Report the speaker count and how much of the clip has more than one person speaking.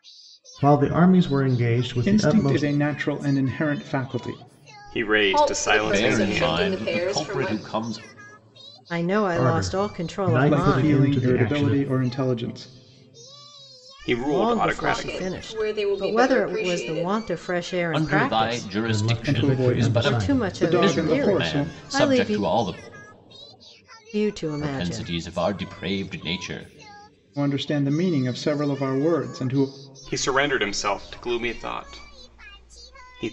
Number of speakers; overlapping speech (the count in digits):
6, about 41%